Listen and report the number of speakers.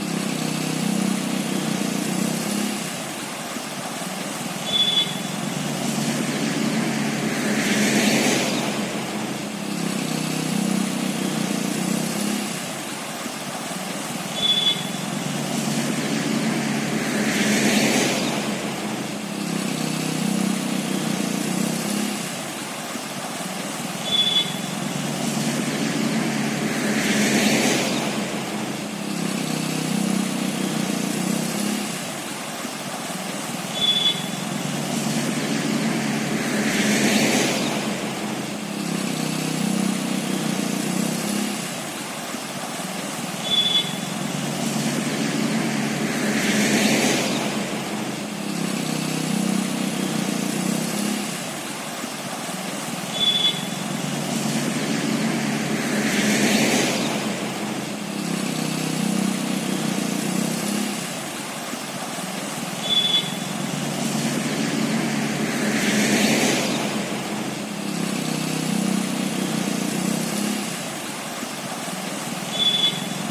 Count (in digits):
0